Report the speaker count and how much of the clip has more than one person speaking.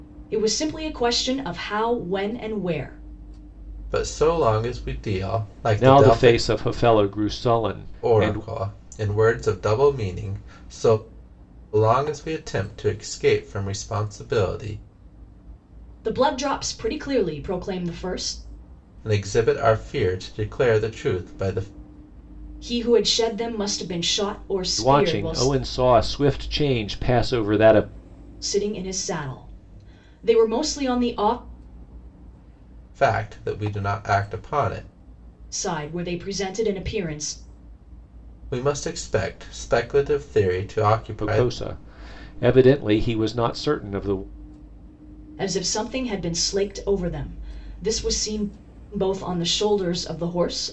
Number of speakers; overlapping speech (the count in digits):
3, about 4%